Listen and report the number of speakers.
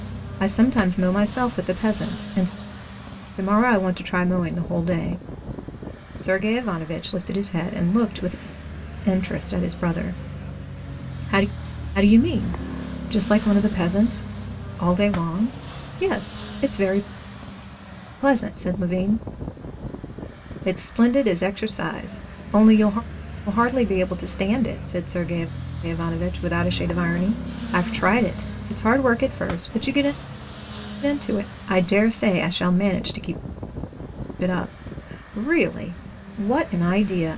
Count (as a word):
one